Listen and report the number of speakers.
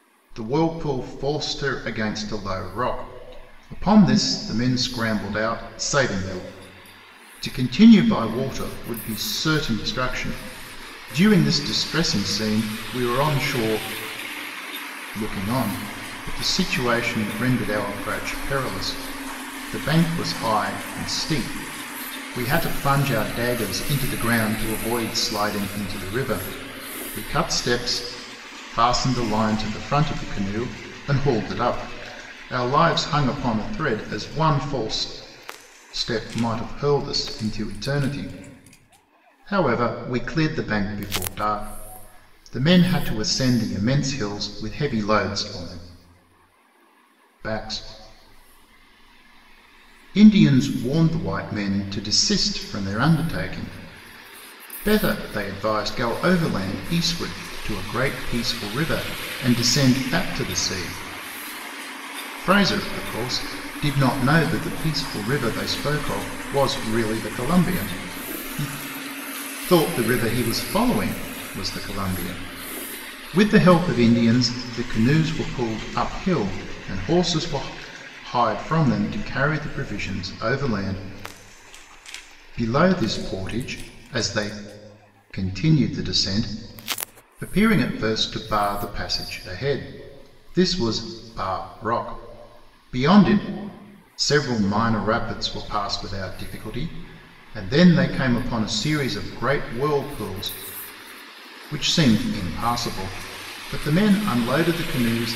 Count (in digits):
1